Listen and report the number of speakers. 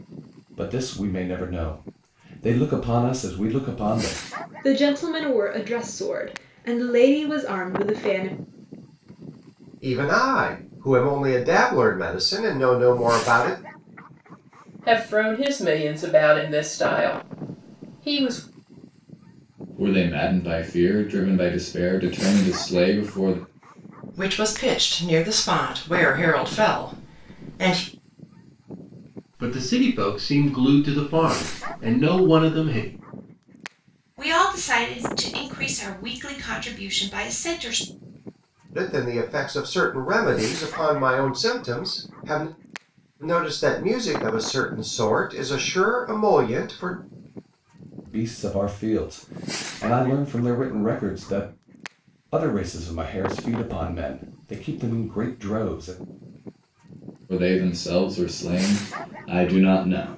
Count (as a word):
eight